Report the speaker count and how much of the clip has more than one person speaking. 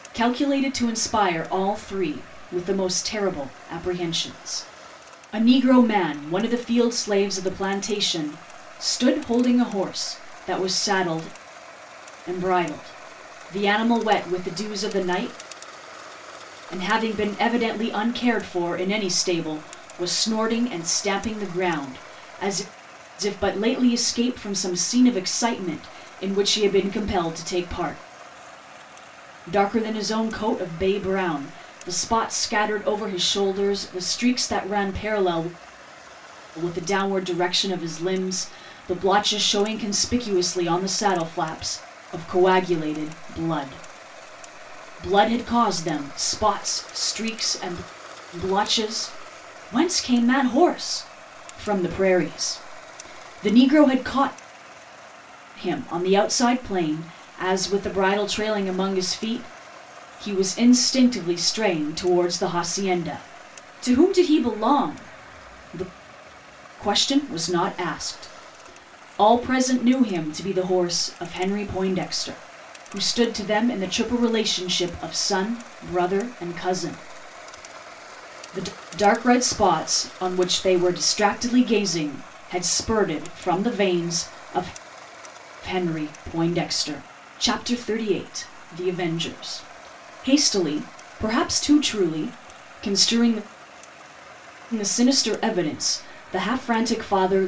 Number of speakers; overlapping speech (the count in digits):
1, no overlap